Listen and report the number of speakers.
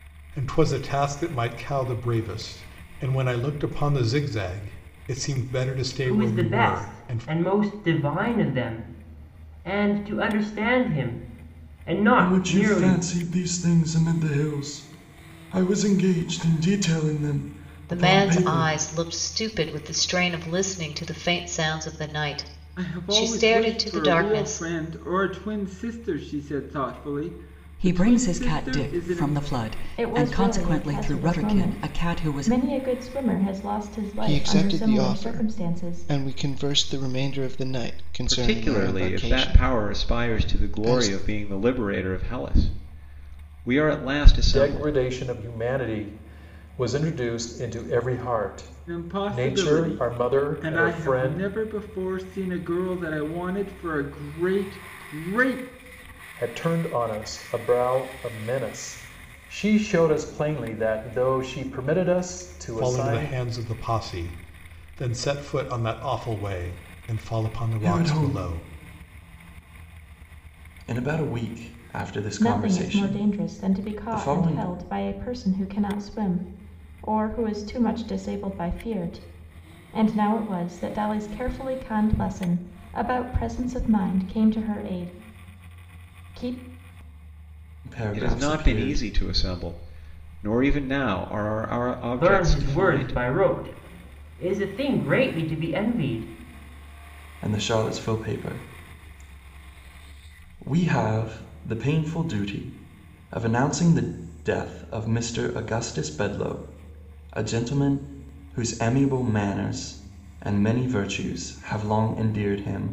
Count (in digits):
10